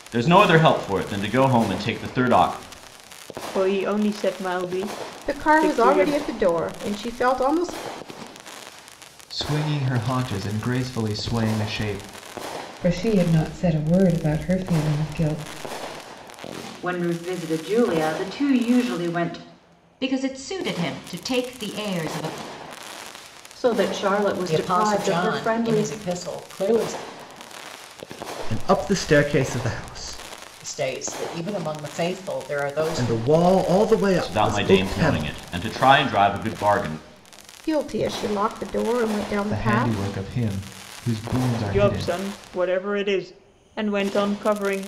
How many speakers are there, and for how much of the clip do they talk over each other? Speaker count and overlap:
10, about 12%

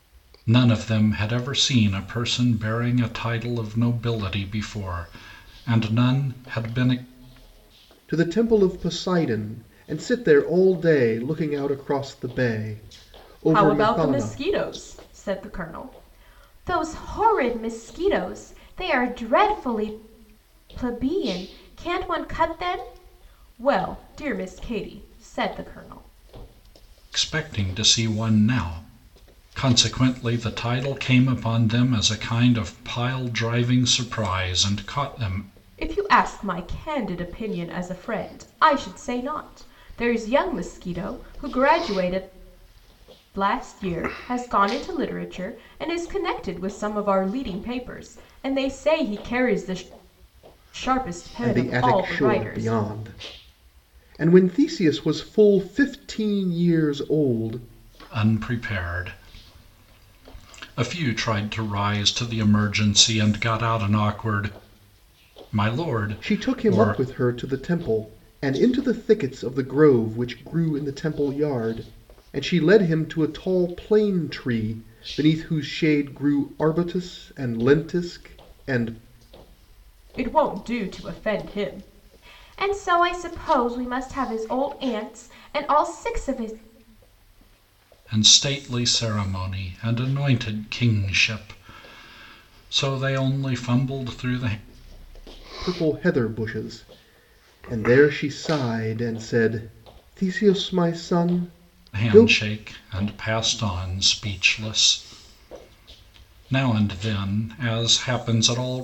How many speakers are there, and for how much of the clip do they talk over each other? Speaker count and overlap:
3, about 3%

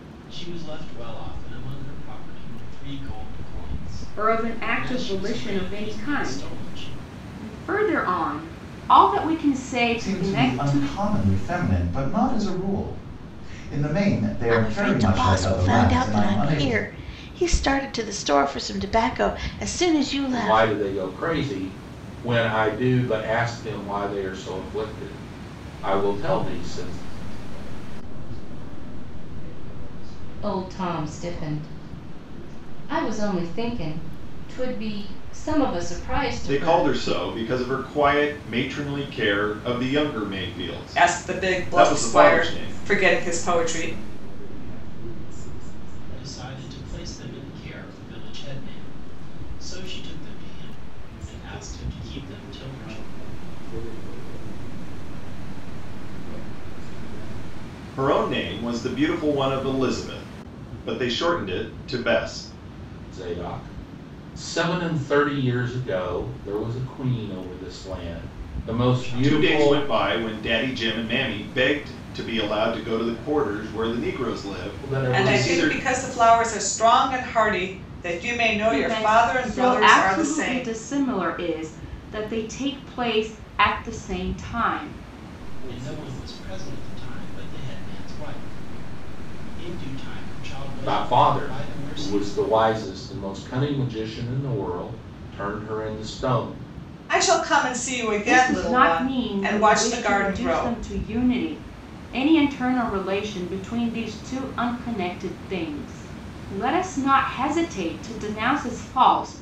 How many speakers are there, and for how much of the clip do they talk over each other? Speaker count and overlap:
10, about 25%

